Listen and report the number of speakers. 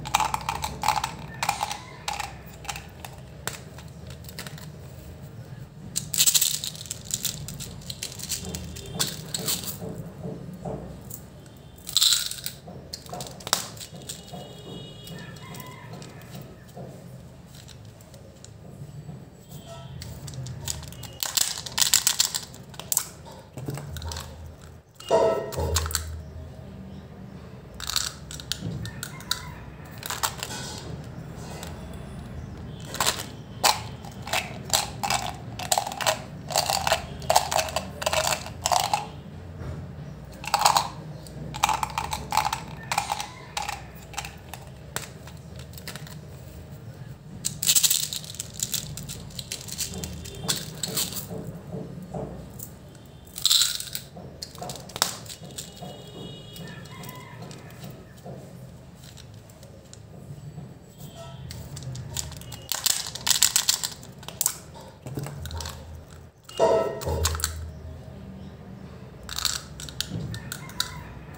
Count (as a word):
zero